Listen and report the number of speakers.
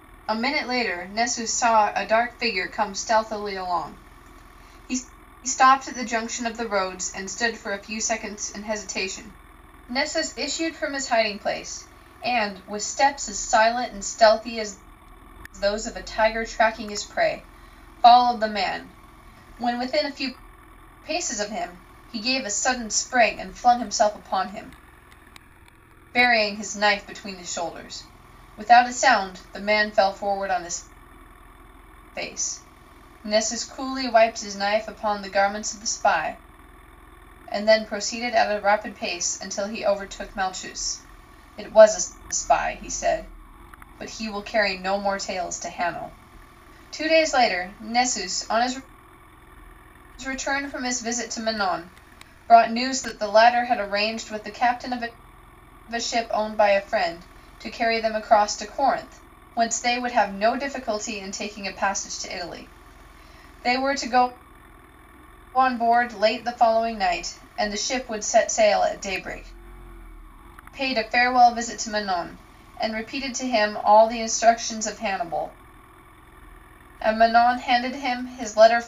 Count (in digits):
1